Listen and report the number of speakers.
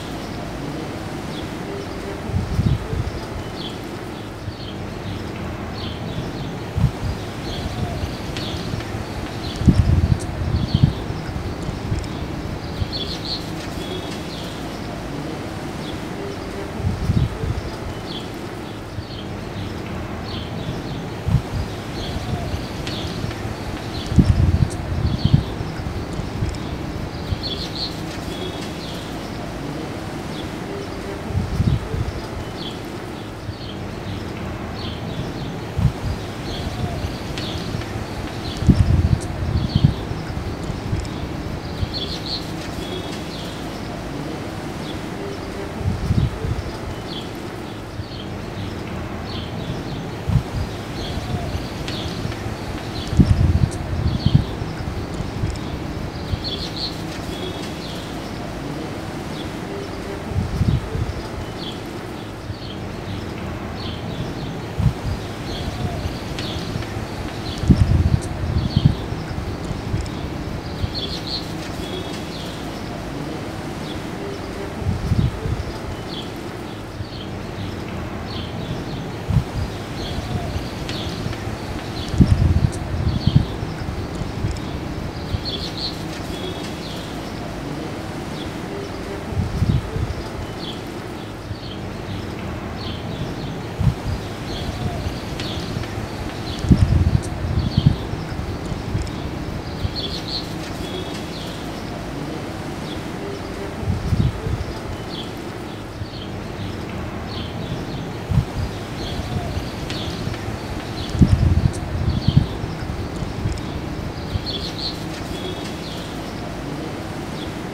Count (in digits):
0